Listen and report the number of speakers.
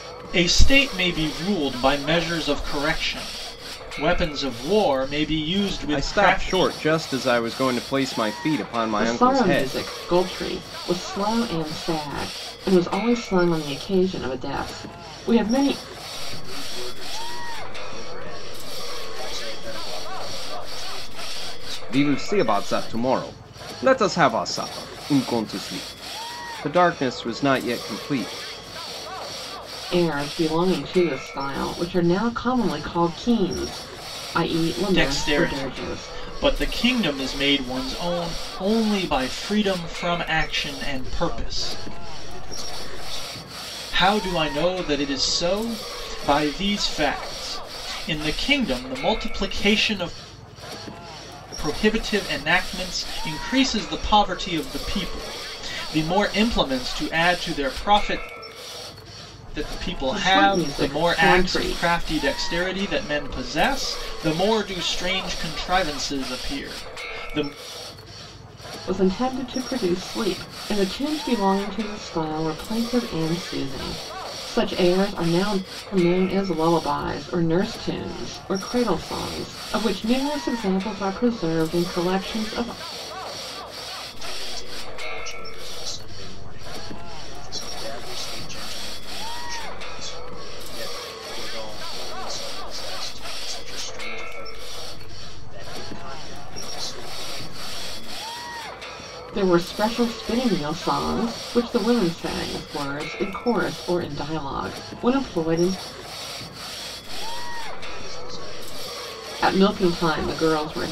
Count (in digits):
4